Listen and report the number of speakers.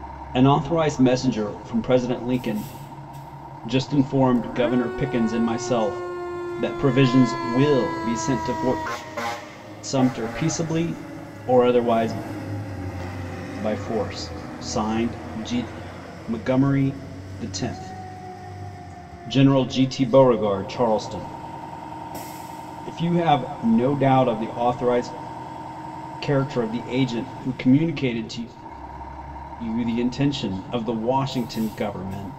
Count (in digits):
1